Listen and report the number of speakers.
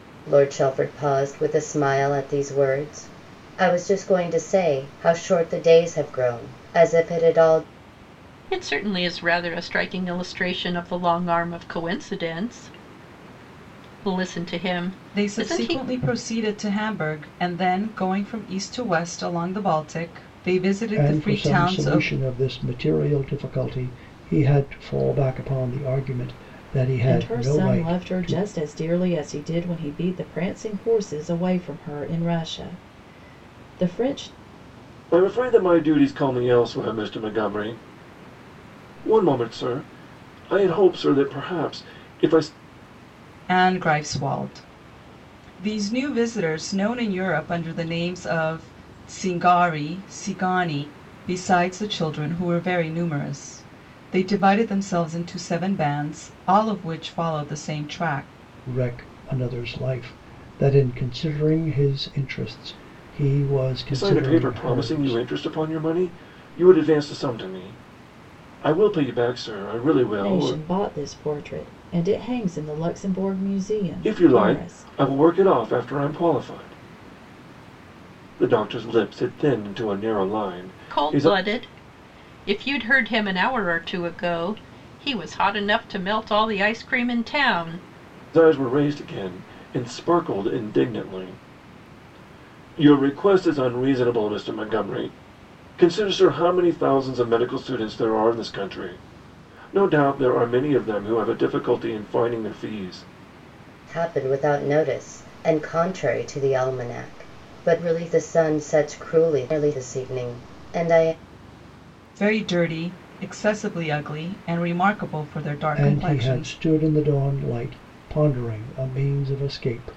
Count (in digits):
6